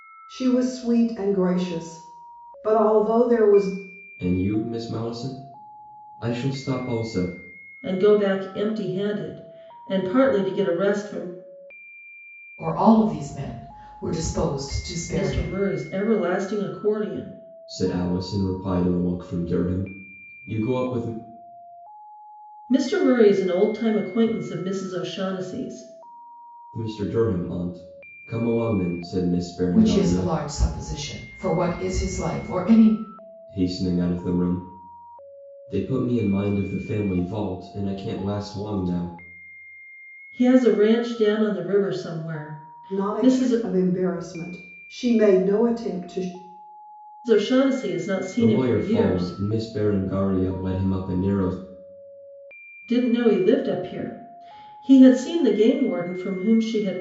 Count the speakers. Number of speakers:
four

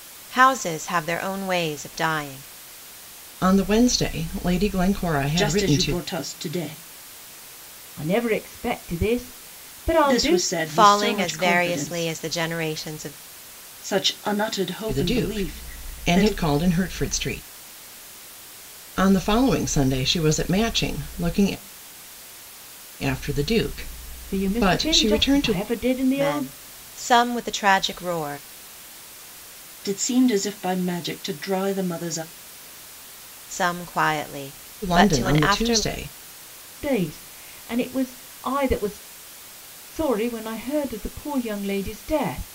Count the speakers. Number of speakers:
four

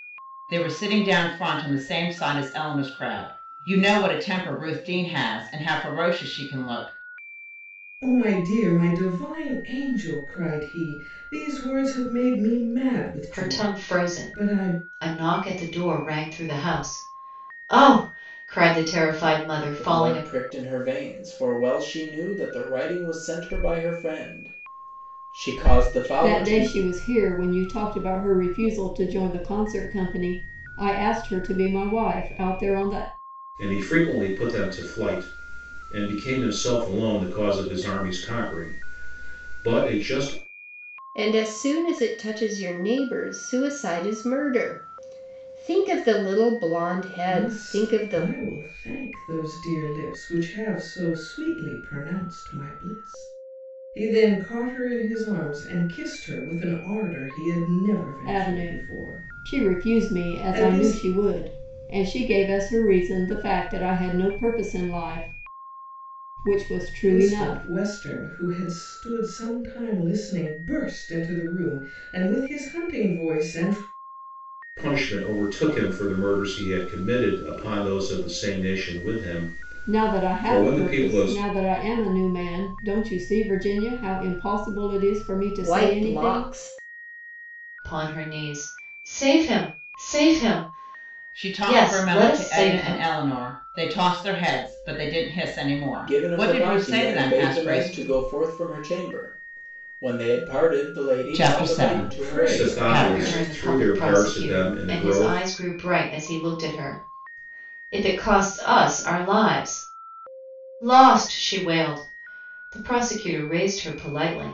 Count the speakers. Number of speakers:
seven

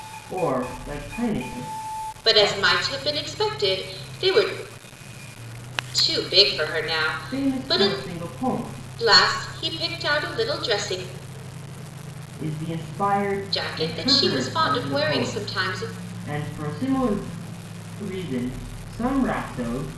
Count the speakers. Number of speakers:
two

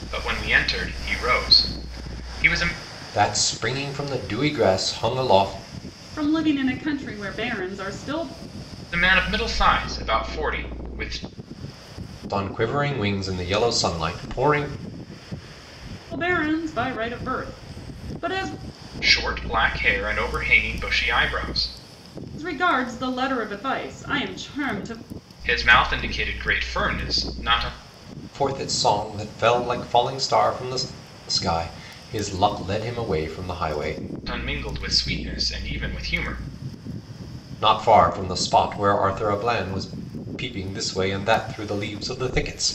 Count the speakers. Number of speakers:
three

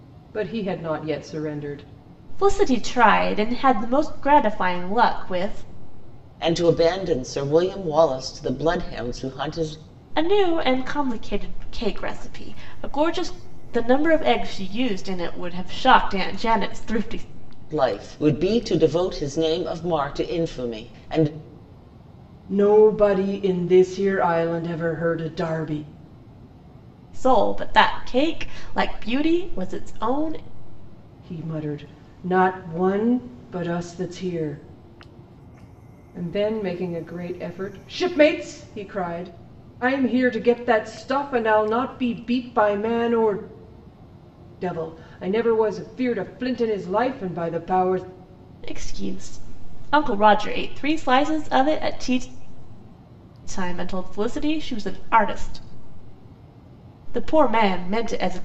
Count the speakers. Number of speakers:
three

